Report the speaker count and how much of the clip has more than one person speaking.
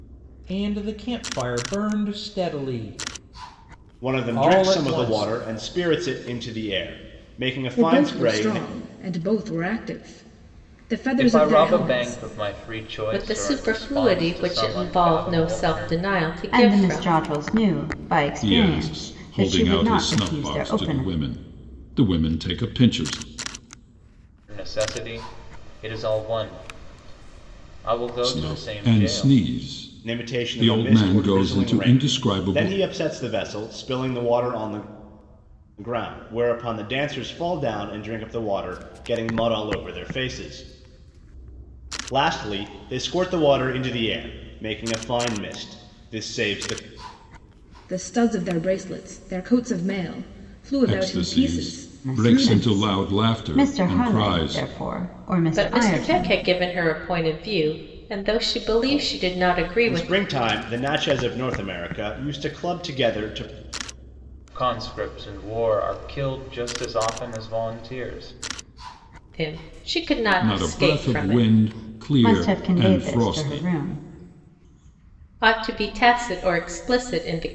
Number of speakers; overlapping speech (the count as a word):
seven, about 29%